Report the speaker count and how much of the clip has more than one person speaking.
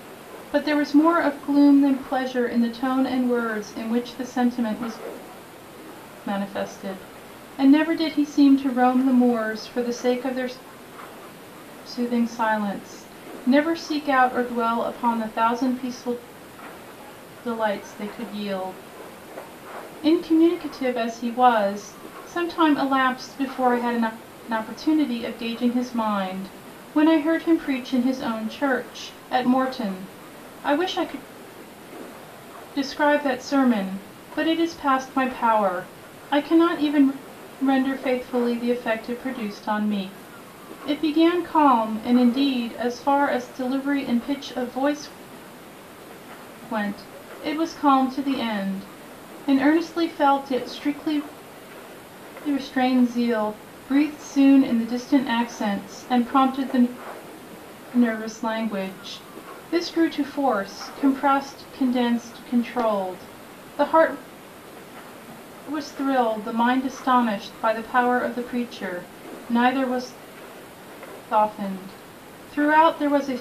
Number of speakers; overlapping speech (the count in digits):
1, no overlap